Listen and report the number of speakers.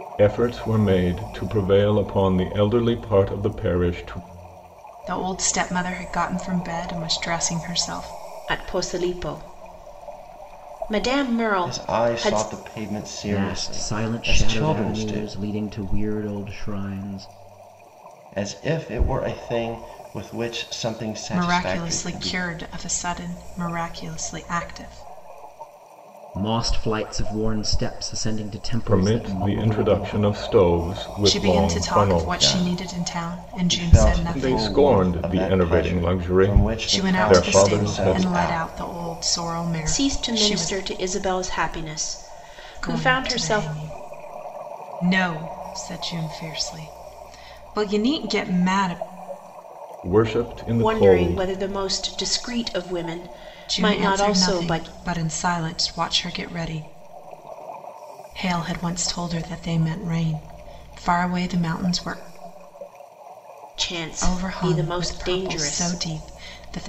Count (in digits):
5